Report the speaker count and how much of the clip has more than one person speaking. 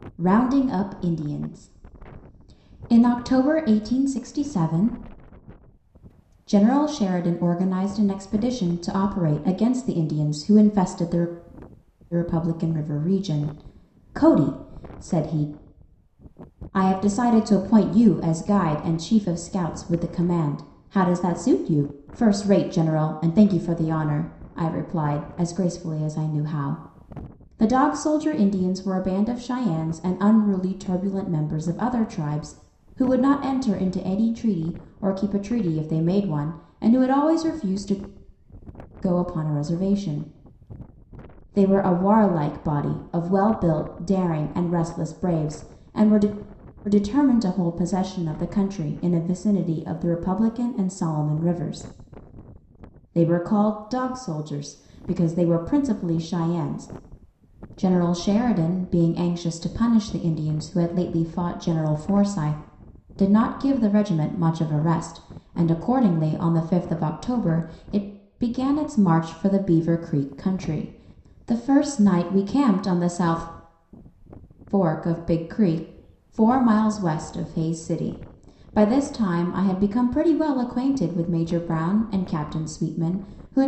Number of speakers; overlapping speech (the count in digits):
1, no overlap